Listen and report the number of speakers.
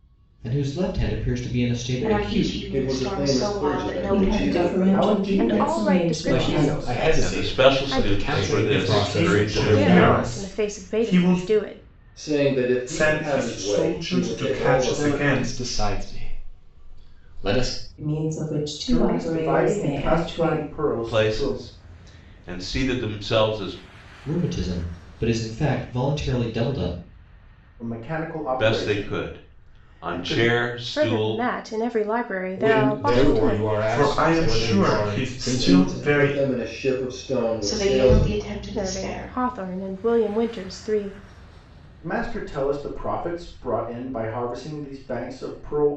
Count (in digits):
10